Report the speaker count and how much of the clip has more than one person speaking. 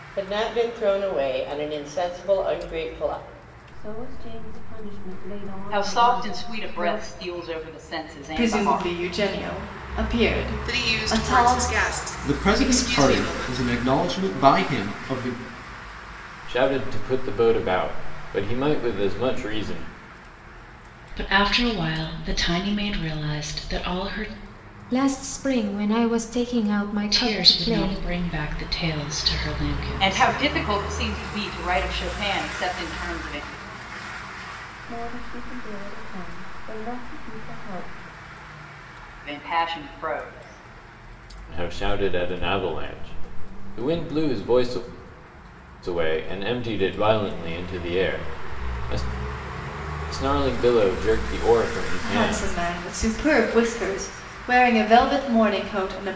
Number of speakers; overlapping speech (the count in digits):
9, about 12%